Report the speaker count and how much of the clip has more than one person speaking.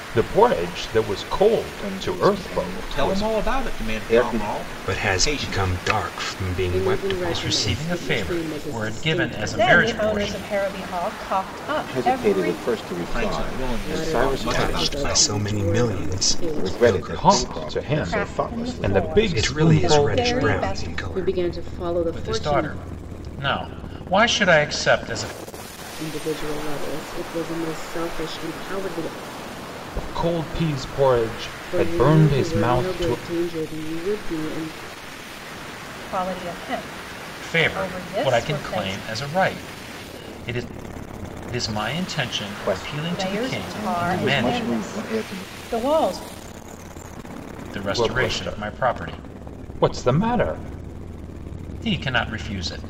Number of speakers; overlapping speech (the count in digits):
7, about 47%